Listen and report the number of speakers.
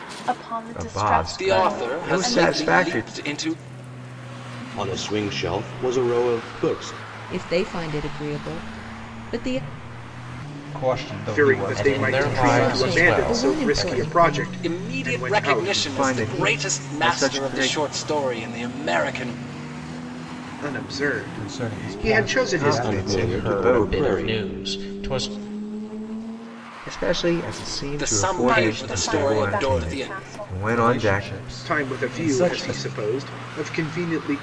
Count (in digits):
8